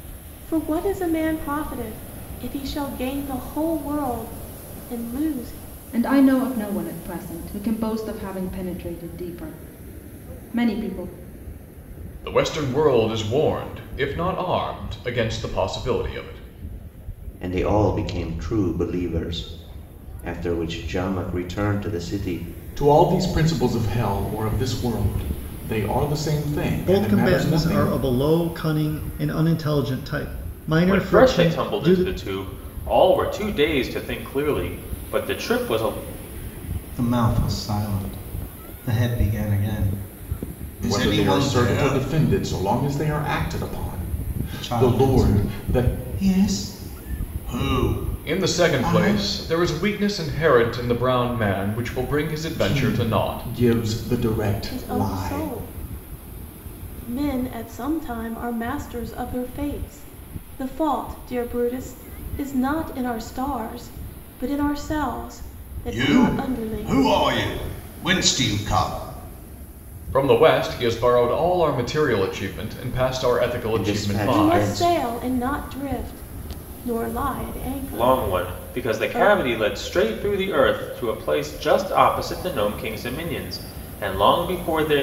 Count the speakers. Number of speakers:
8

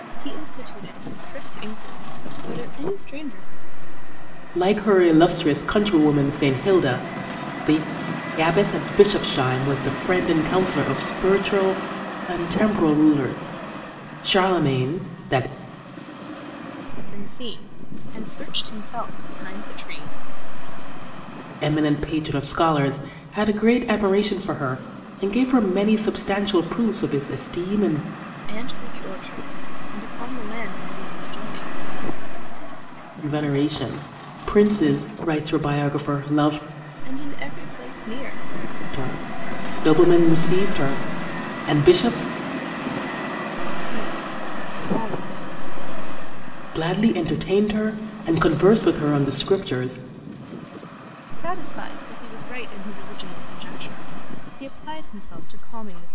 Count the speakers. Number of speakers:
2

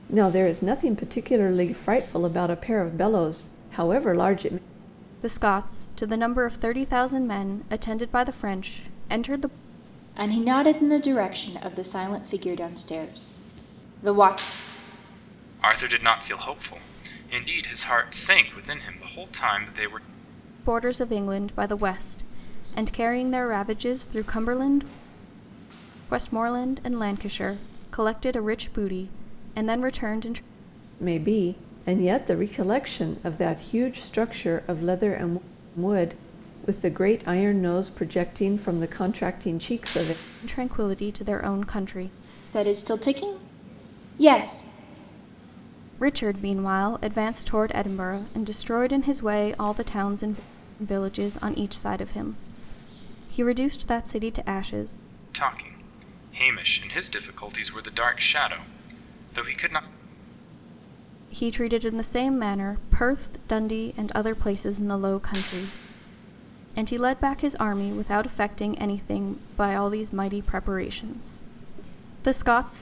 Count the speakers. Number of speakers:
4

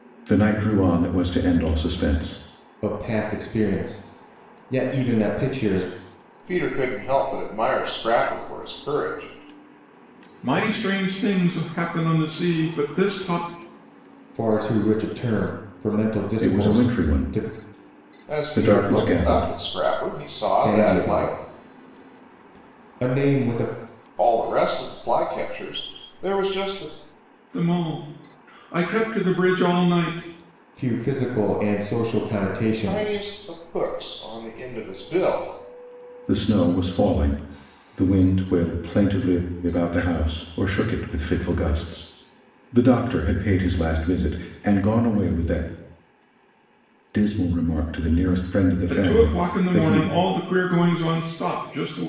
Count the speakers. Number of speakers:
4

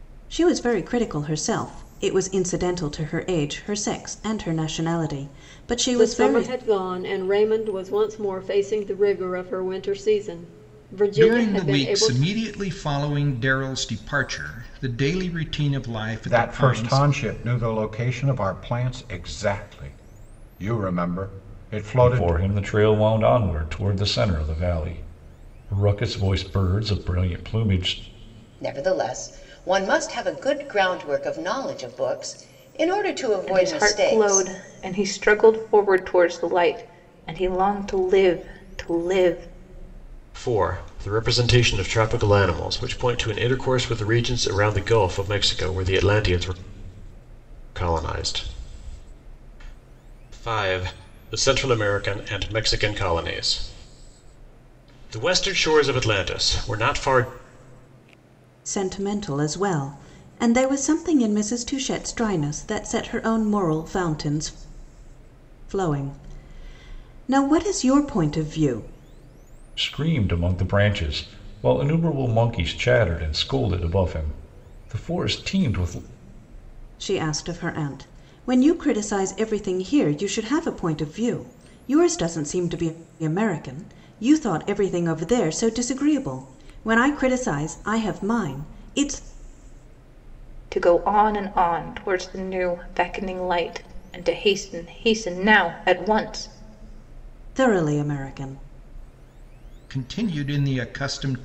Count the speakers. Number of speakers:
8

